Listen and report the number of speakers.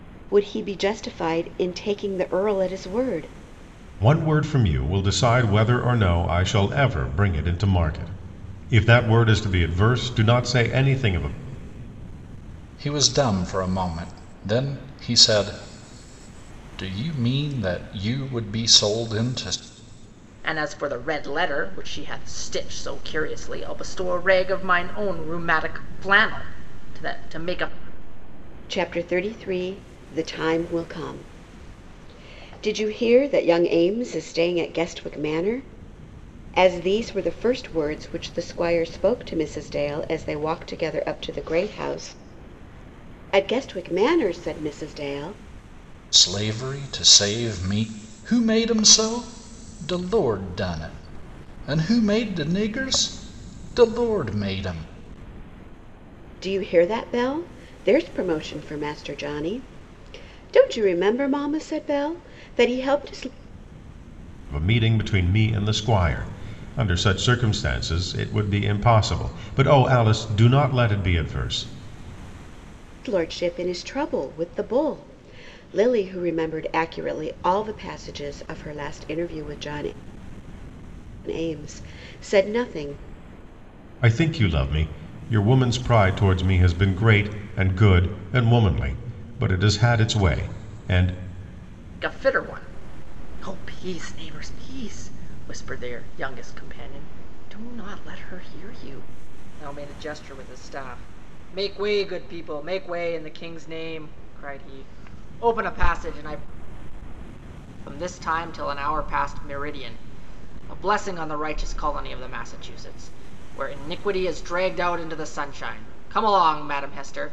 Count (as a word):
four